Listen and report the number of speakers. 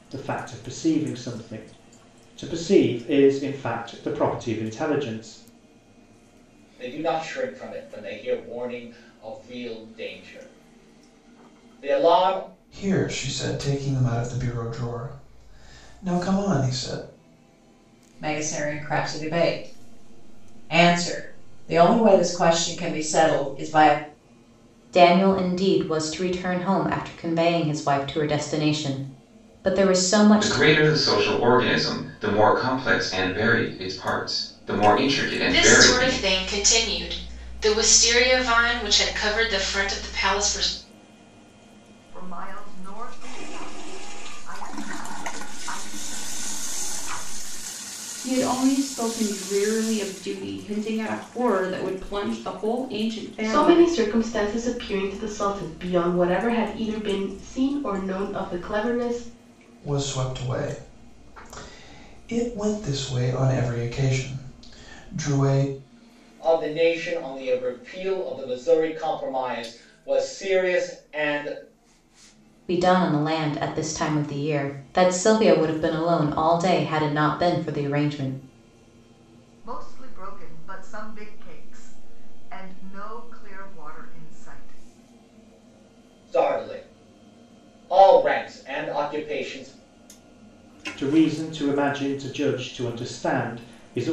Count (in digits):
10